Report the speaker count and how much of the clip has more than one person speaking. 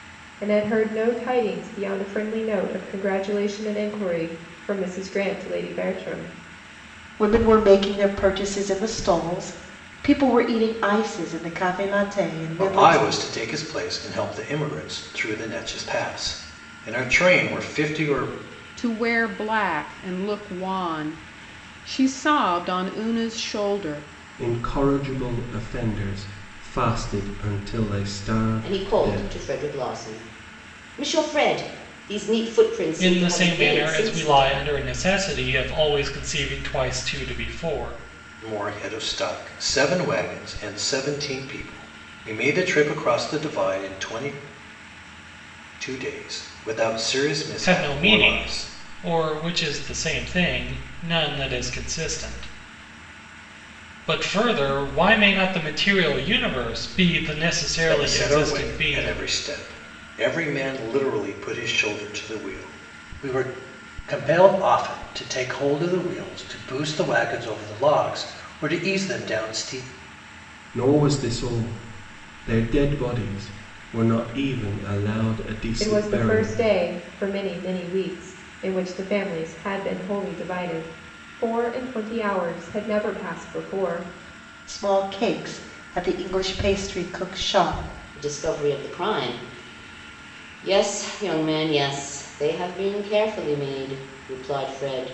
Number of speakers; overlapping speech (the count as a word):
seven, about 7%